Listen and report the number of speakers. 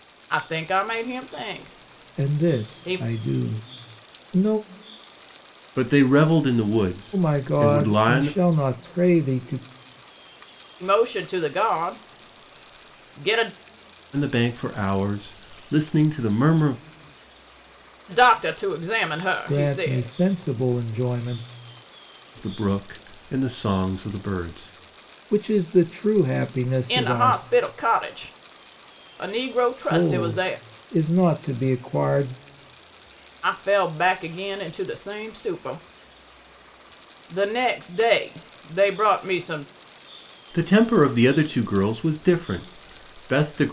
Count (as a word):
three